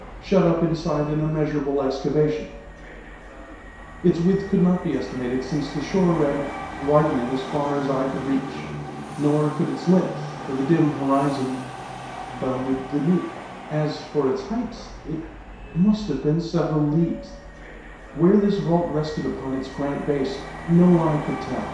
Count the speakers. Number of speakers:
one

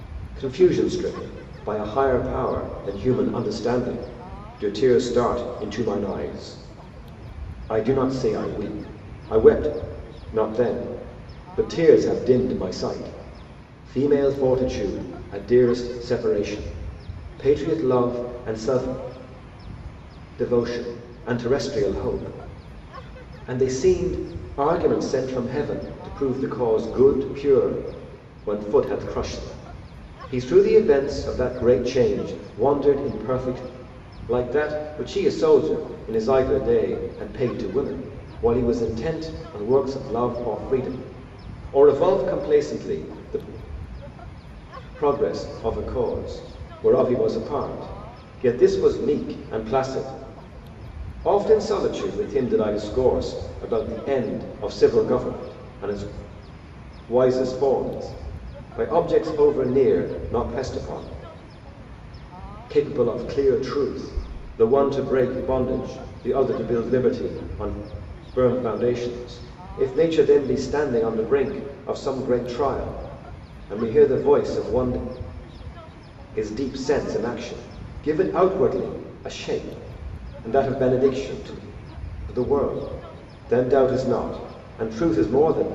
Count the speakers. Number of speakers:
one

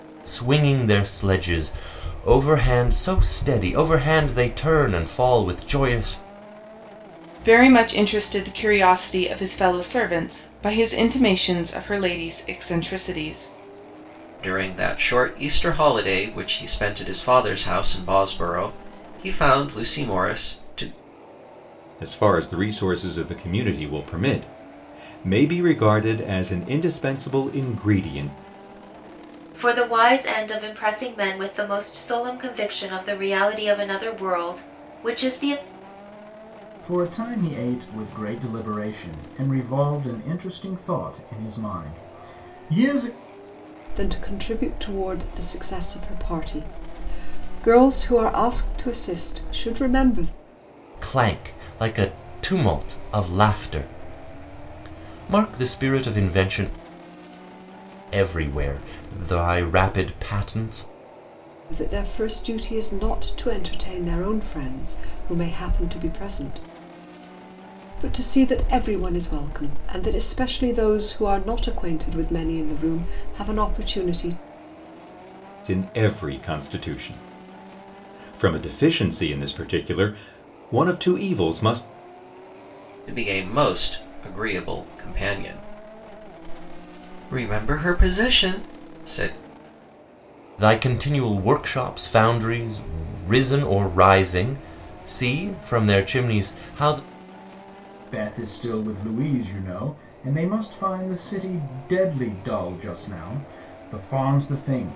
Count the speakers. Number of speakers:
seven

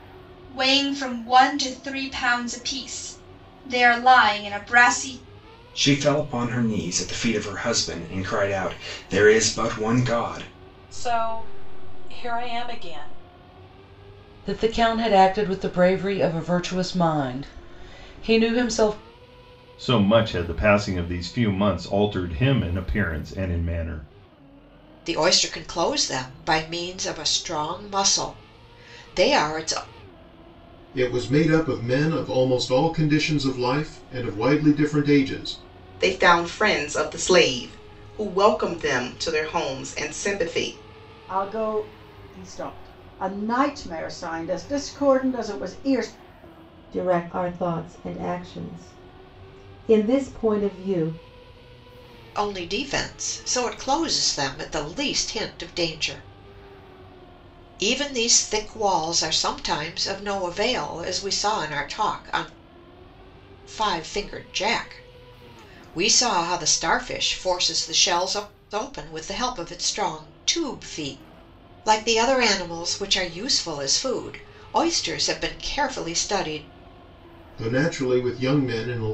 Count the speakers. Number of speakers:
ten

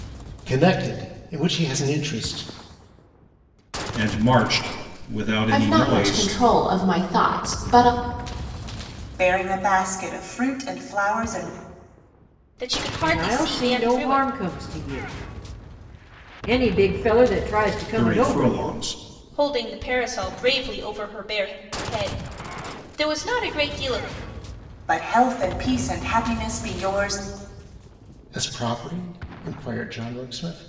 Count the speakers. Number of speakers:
six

